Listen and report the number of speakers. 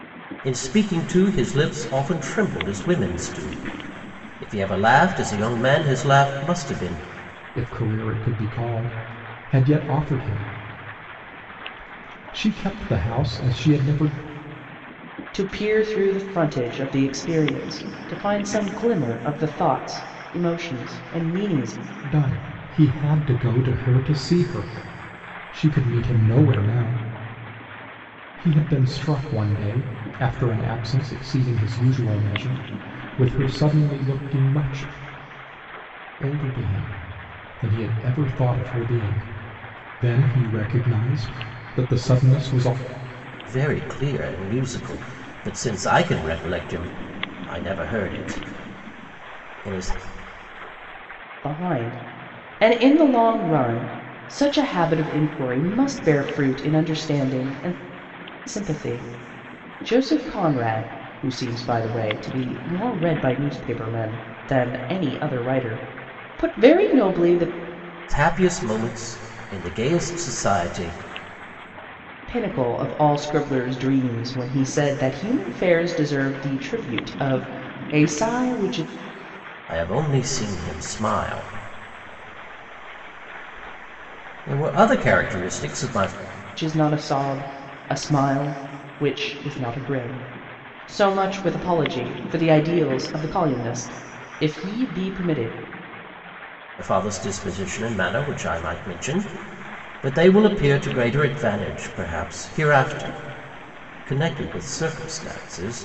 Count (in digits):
3